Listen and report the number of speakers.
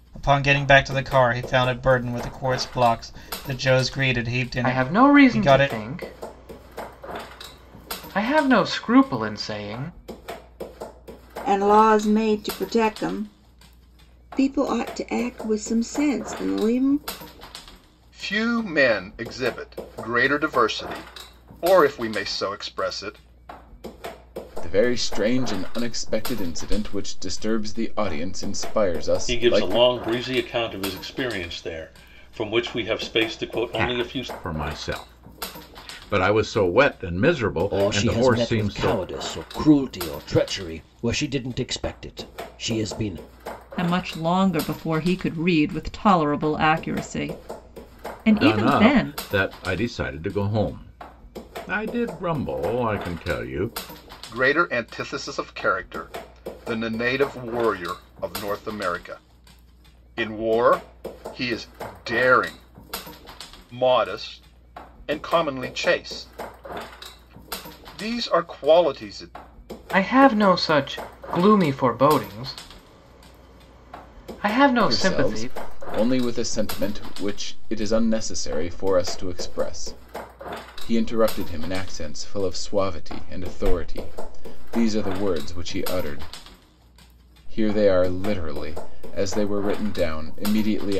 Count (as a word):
nine